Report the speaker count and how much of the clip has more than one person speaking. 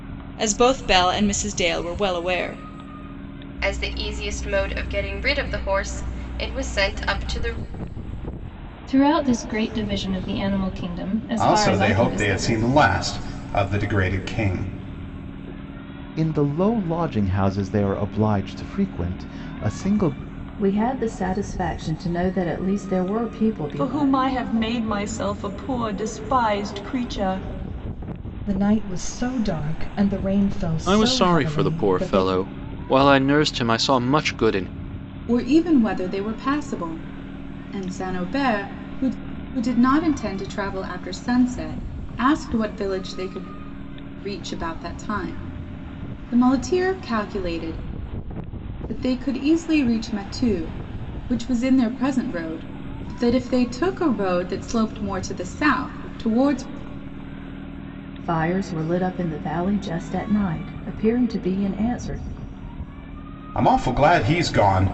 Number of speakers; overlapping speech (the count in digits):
10, about 5%